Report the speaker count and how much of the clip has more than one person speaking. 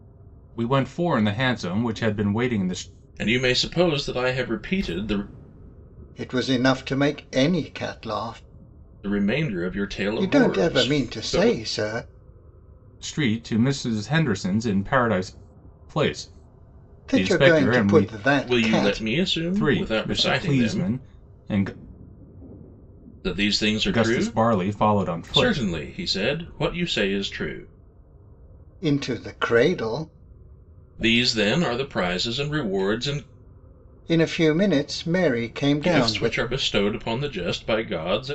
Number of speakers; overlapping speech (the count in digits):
3, about 16%